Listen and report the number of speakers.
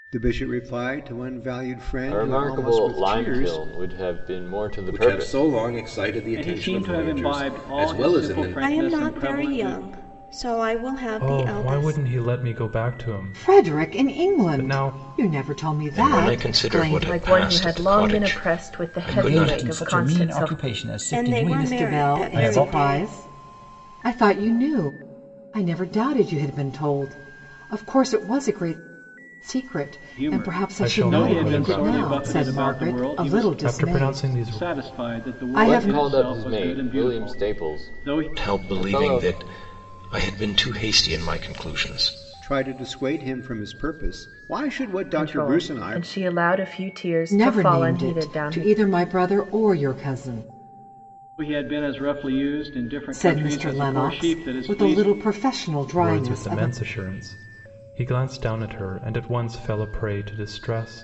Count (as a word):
ten